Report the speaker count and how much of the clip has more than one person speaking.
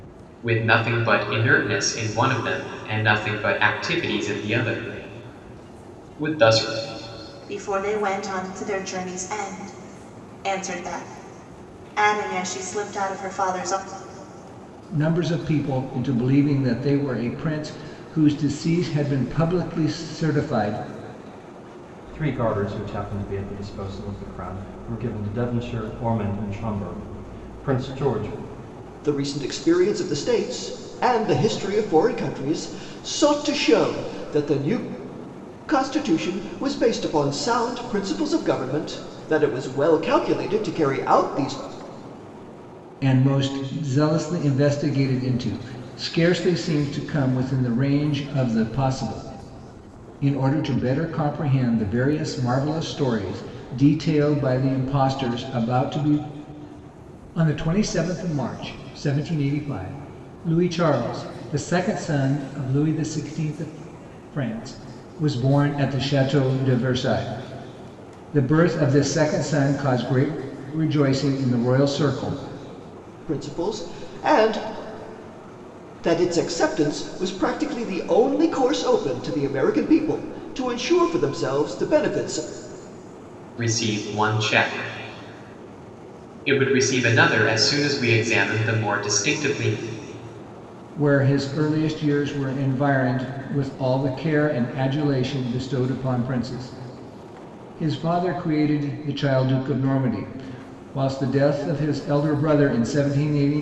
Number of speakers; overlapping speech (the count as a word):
five, no overlap